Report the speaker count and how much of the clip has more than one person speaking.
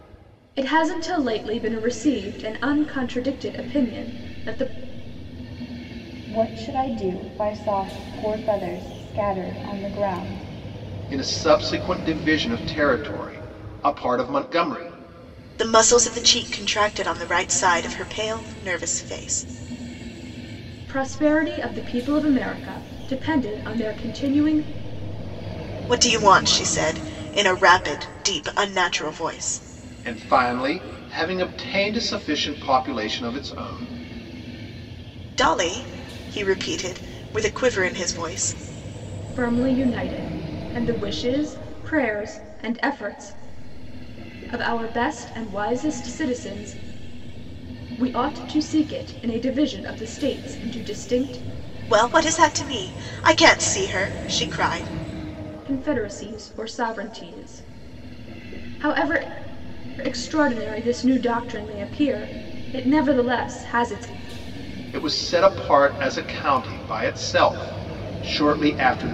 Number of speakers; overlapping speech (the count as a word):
four, no overlap